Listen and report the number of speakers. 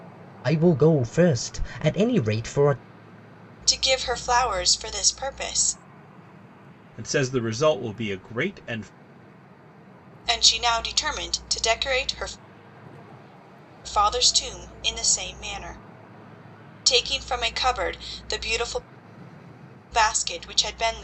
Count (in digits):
3